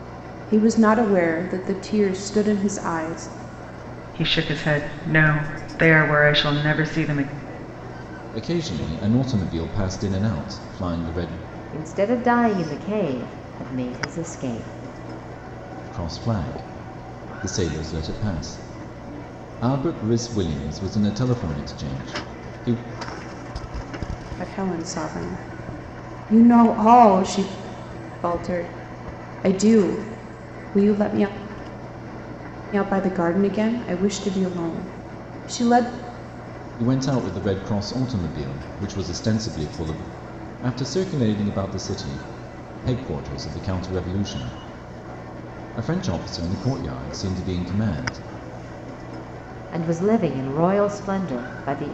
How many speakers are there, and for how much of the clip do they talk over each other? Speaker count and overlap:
four, no overlap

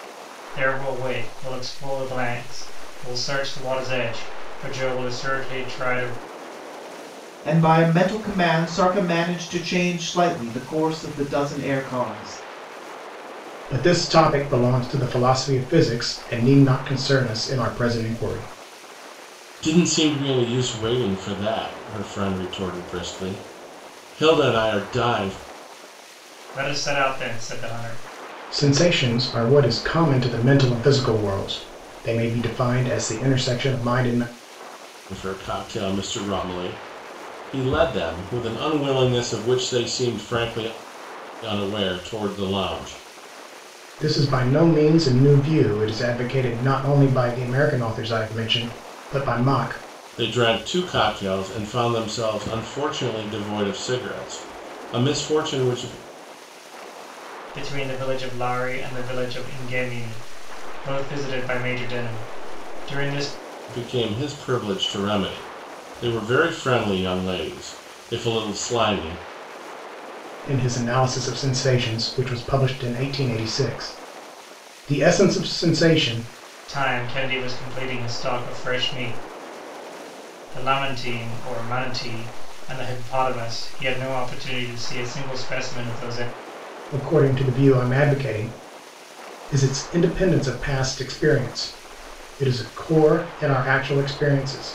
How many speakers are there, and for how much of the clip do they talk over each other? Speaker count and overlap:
four, no overlap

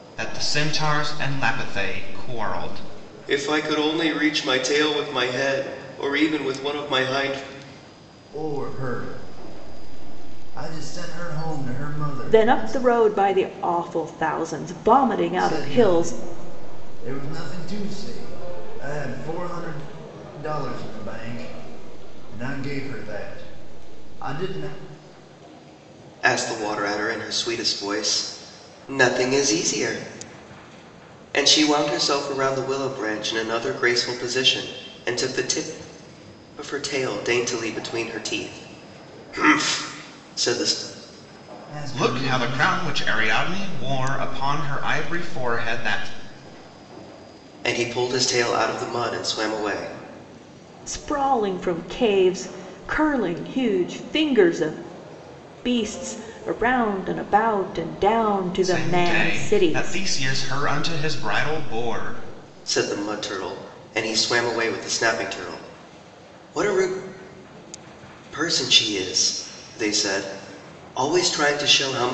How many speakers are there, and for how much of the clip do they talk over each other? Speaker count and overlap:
four, about 5%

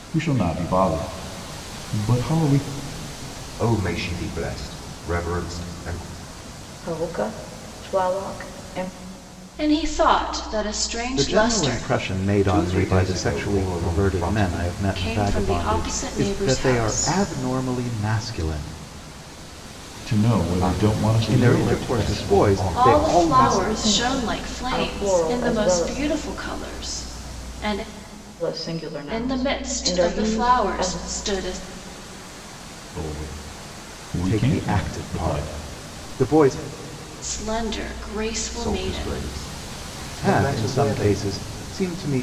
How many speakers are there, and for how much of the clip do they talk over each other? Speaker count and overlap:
five, about 37%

